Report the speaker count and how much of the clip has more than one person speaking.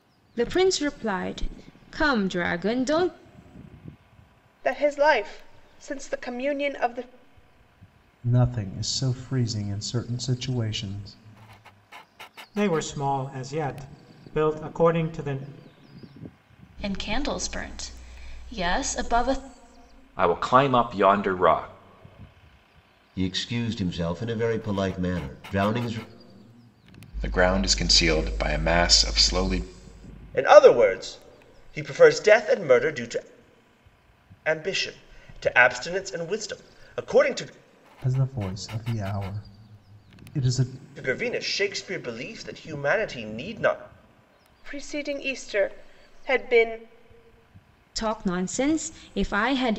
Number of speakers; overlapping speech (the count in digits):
9, no overlap